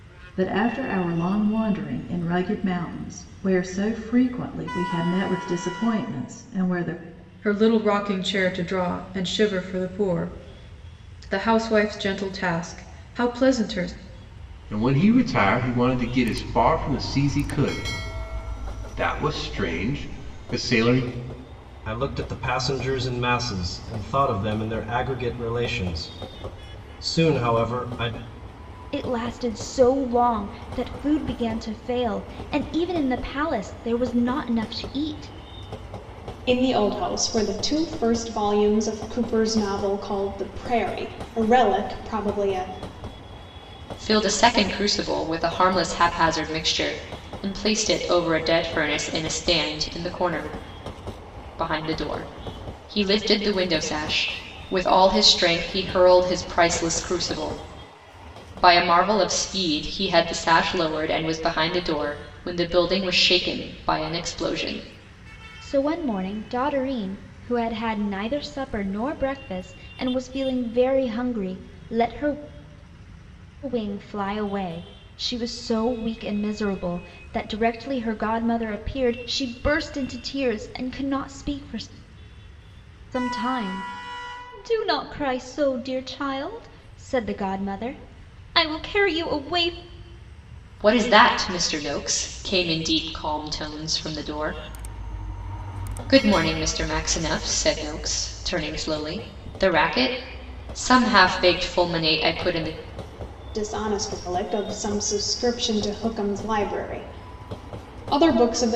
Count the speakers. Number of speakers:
seven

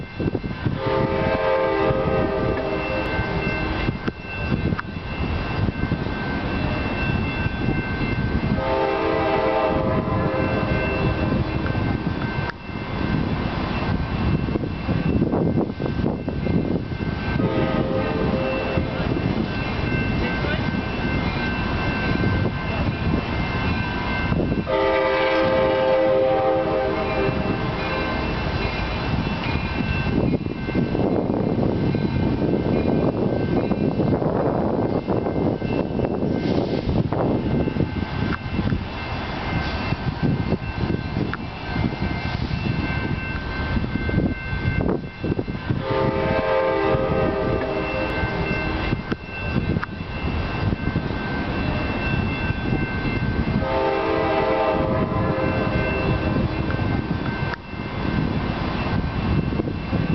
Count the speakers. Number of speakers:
zero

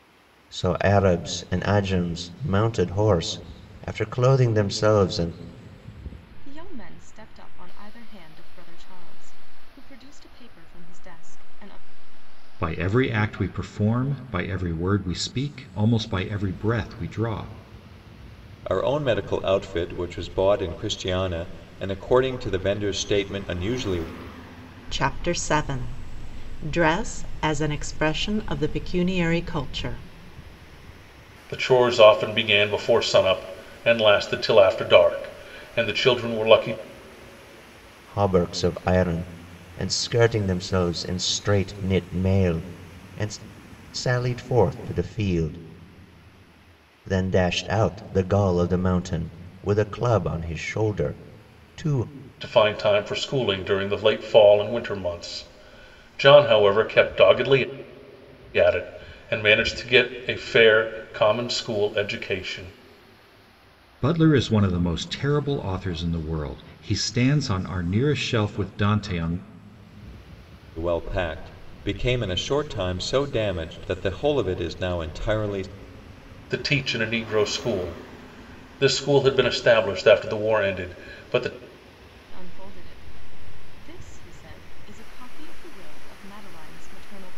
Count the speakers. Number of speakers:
six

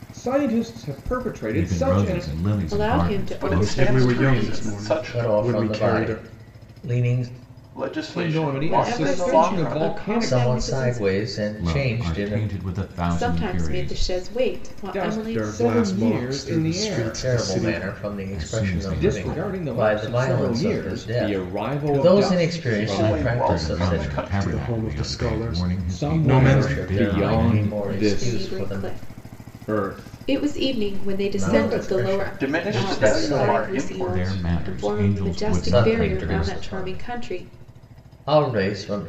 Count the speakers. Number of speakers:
six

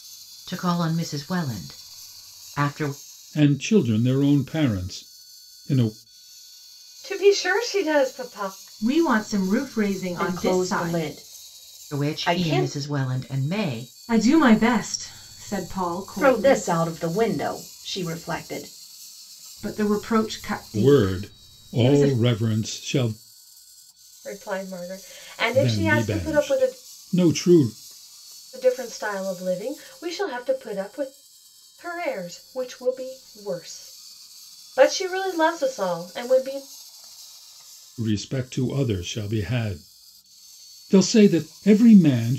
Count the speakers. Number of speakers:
five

